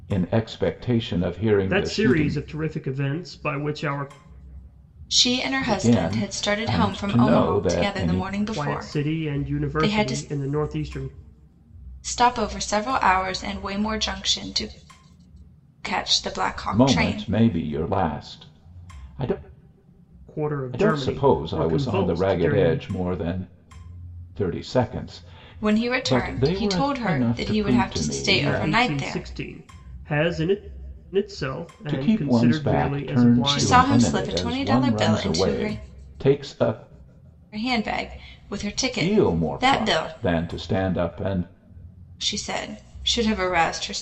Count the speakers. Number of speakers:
3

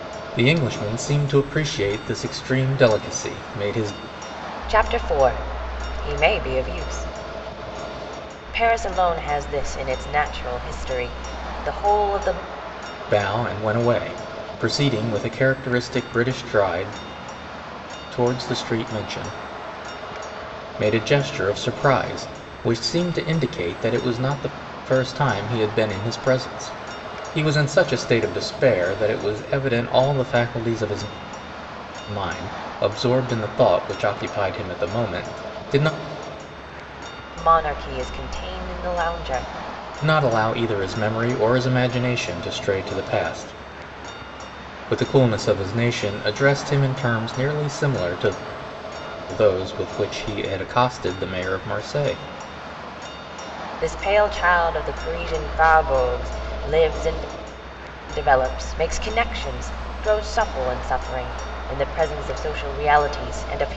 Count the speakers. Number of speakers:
2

